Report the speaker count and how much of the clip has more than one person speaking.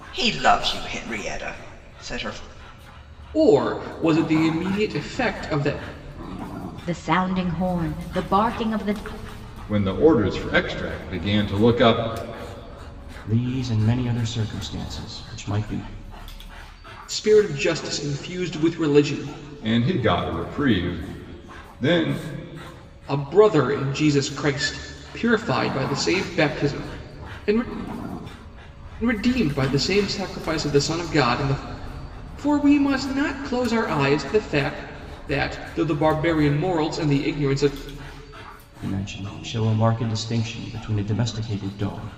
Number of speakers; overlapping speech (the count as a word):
five, no overlap